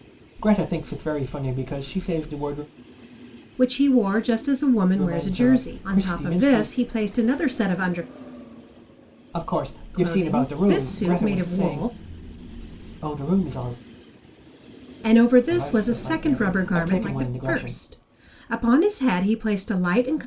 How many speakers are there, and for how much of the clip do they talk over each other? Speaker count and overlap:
2, about 31%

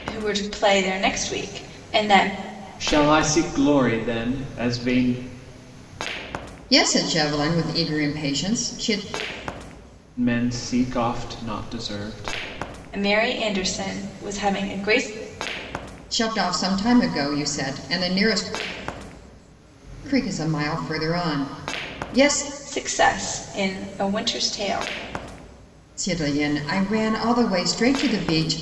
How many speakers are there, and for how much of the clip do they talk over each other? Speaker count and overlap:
3, no overlap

